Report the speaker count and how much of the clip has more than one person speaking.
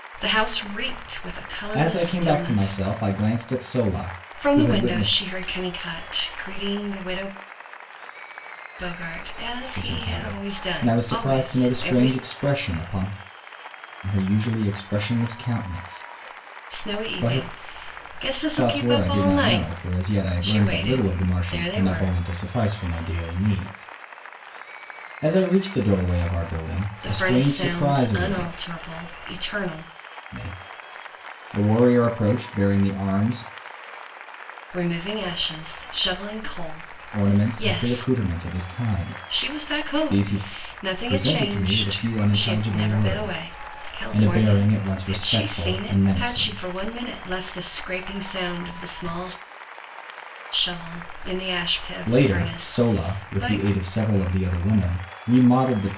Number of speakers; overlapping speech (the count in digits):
2, about 33%